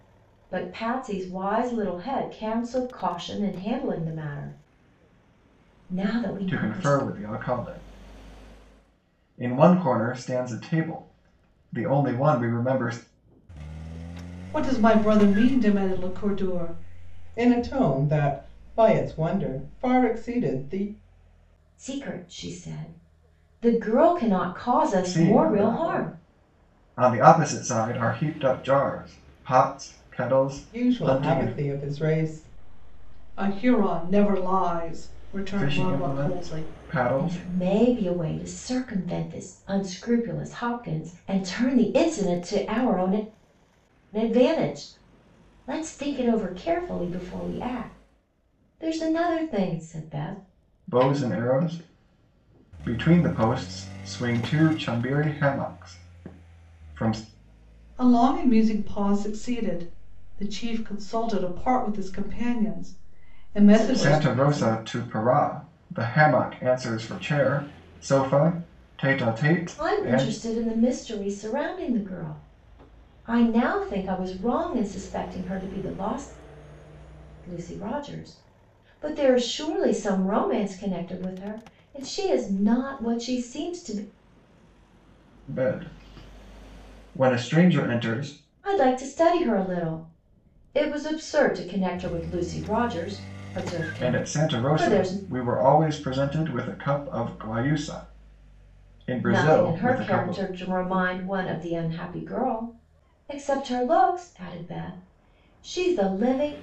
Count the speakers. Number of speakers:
three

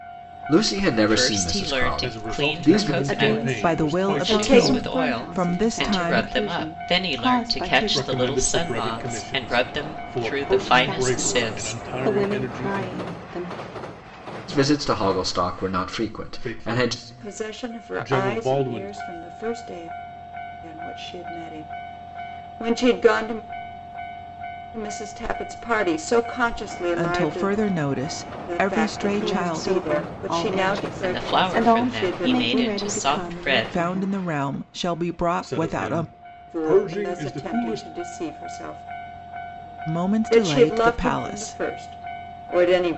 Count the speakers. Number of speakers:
six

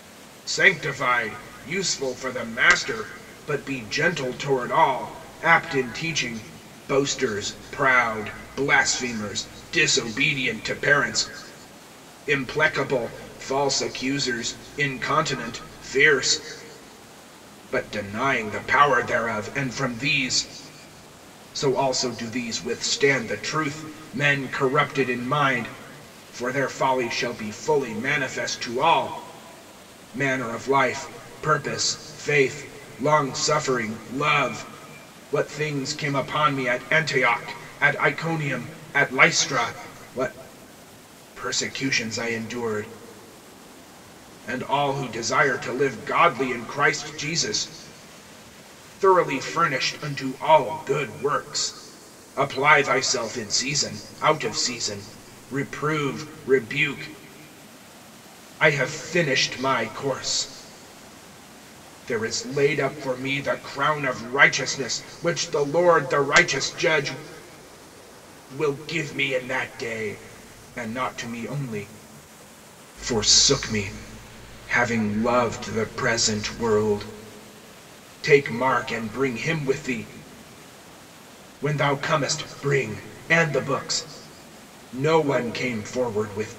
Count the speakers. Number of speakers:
one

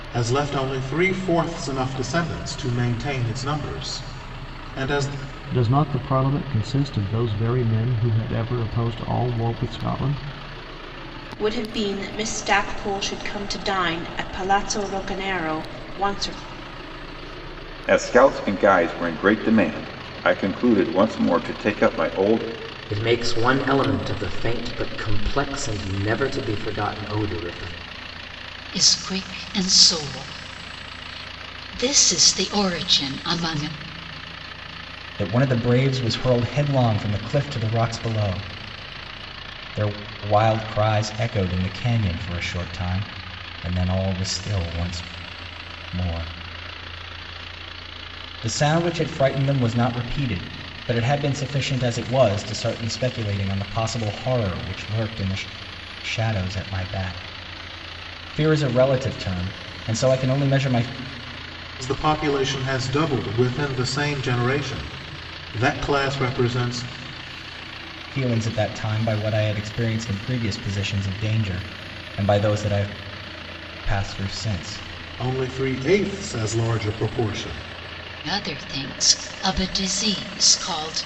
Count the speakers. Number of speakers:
seven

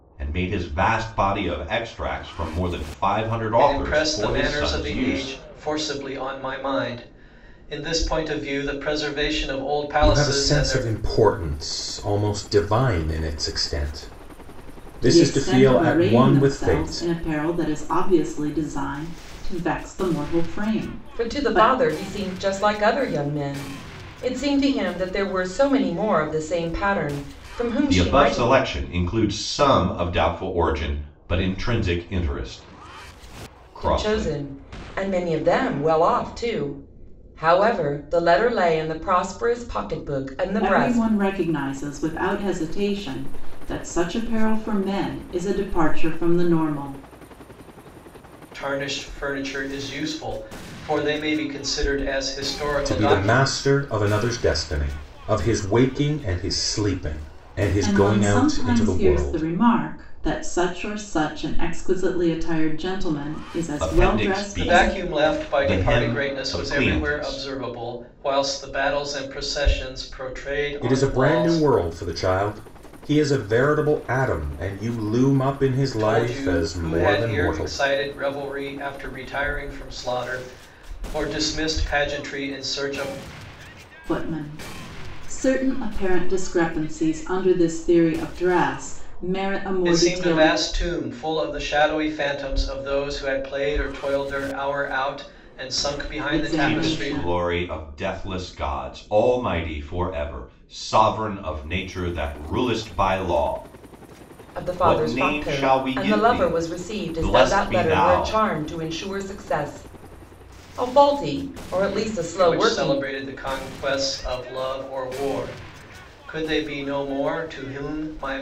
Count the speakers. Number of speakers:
five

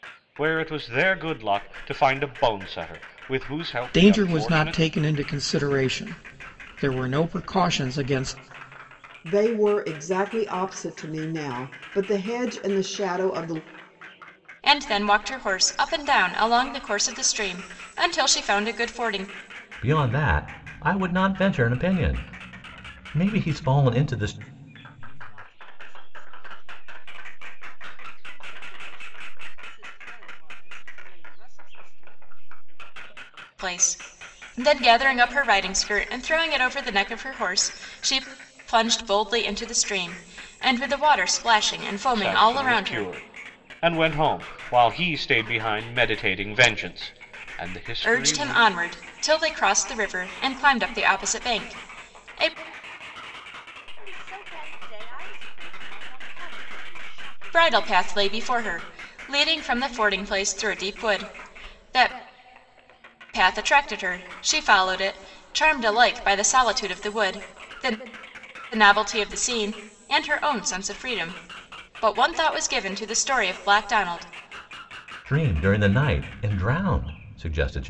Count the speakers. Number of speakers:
six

